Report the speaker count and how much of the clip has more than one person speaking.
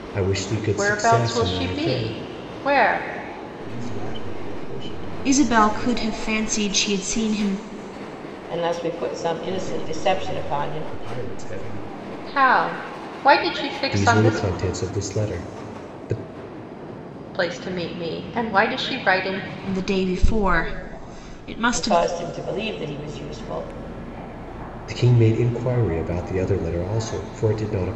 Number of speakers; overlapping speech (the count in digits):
5, about 18%